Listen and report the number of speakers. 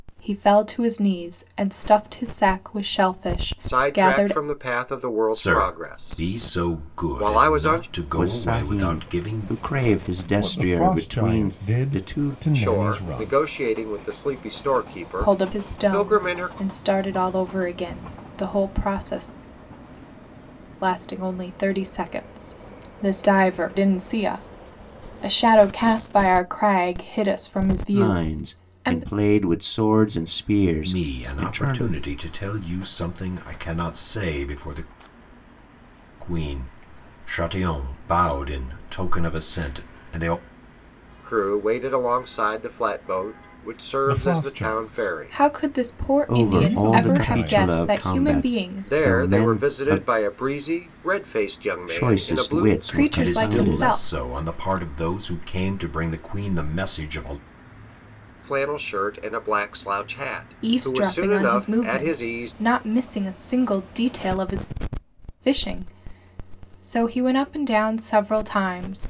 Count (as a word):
five